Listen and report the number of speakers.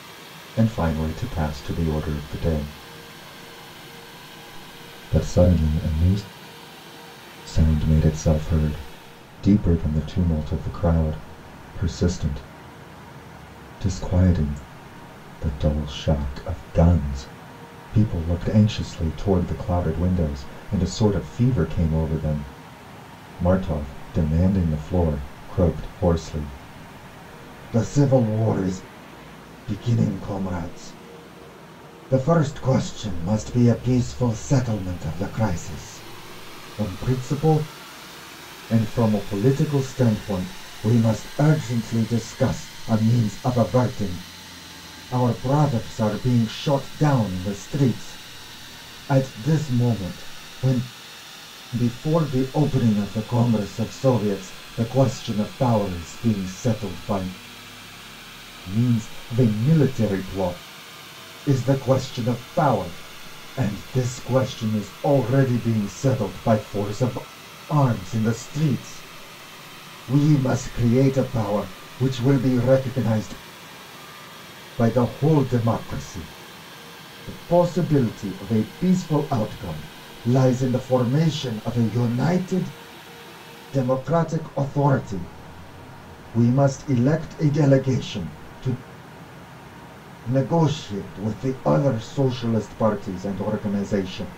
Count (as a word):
one